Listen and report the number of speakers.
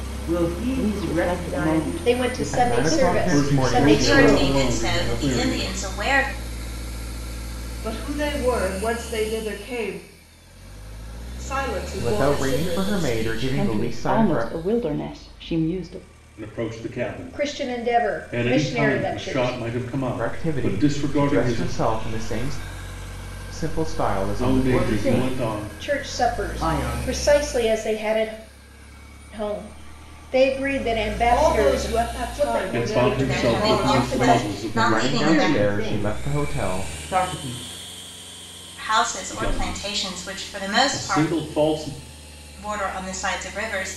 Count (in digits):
7